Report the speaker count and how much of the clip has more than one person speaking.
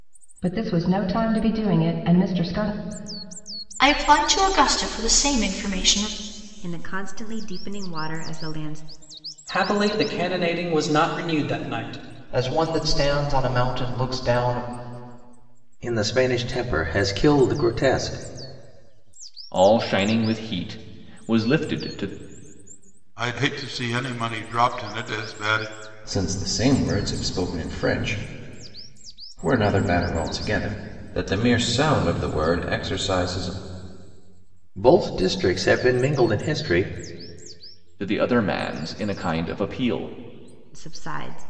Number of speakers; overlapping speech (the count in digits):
9, no overlap